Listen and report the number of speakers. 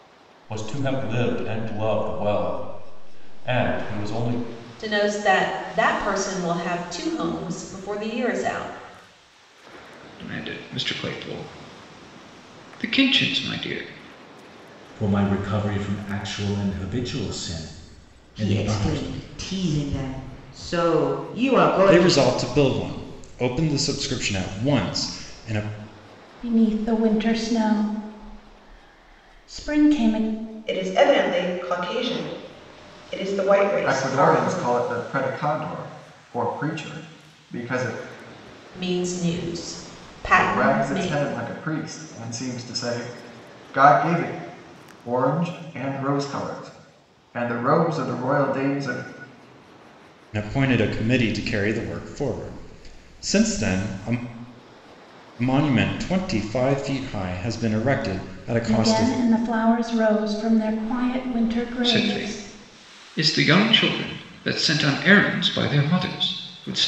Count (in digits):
9